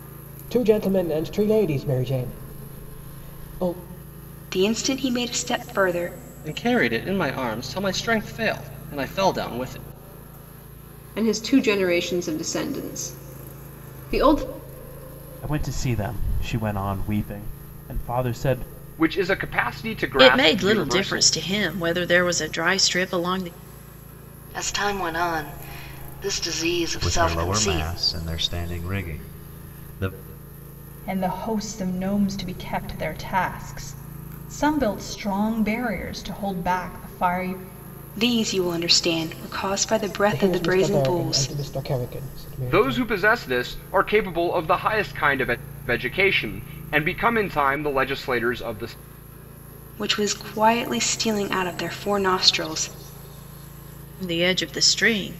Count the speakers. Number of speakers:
10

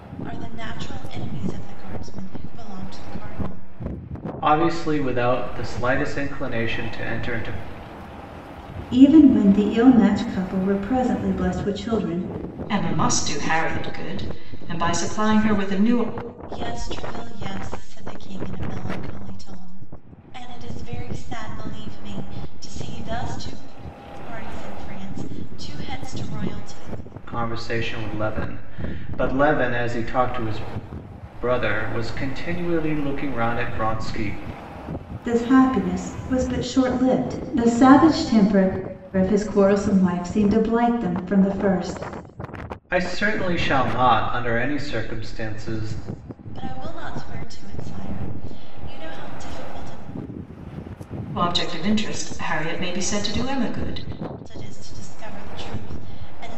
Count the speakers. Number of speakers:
4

